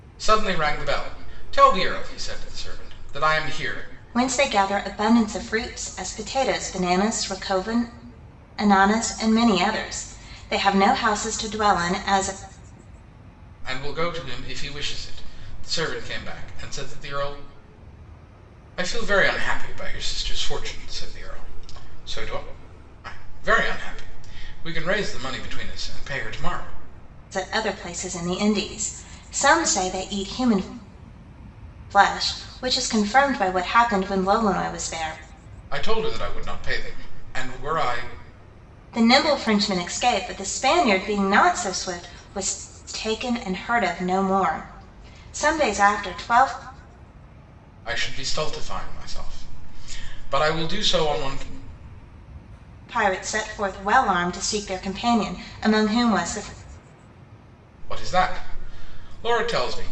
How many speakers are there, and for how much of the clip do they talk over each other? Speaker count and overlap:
2, no overlap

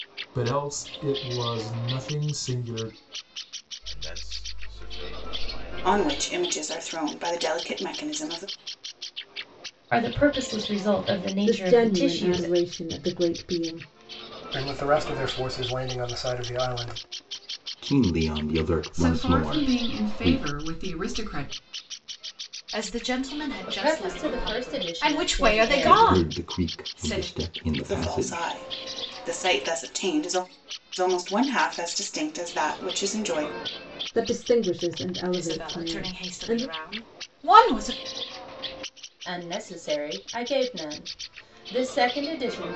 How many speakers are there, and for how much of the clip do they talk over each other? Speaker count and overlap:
10, about 20%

